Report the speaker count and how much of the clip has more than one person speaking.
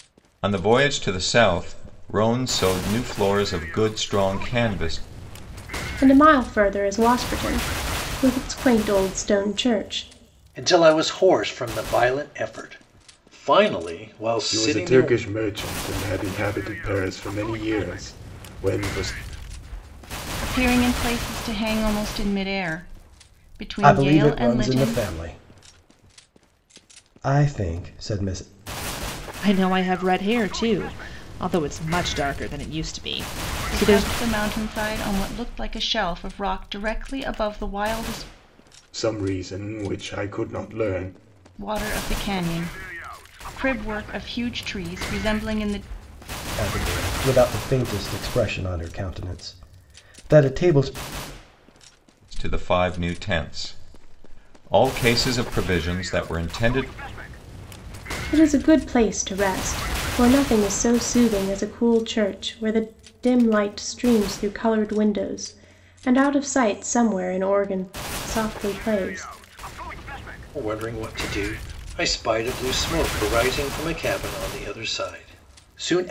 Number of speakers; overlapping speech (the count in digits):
7, about 3%